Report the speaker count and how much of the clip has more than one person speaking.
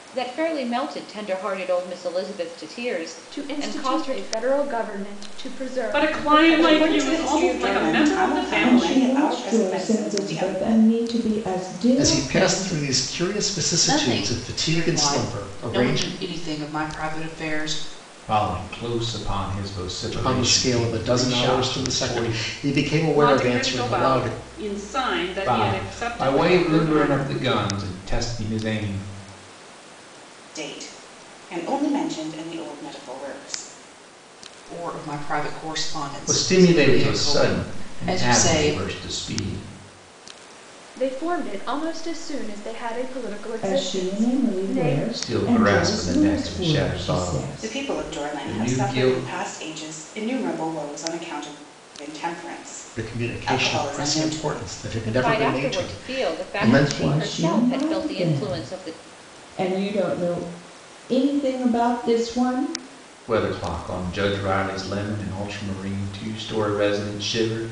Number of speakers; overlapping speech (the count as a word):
eight, about 42%